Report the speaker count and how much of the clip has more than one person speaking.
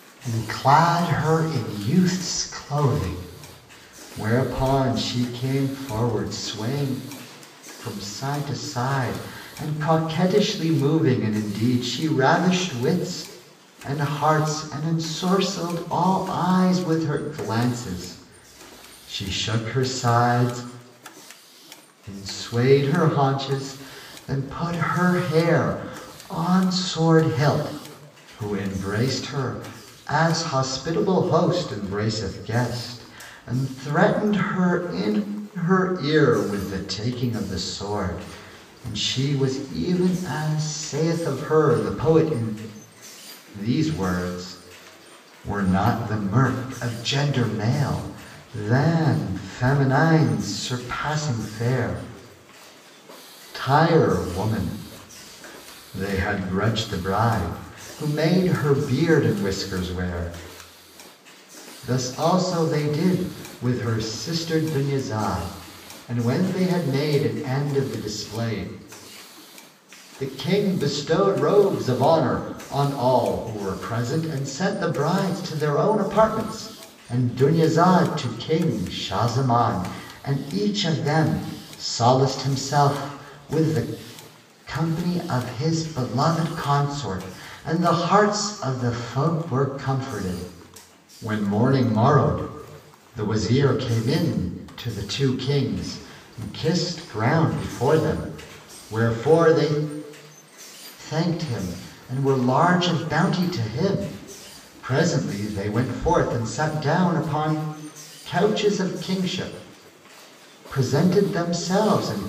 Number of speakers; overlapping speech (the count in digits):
1, no overlap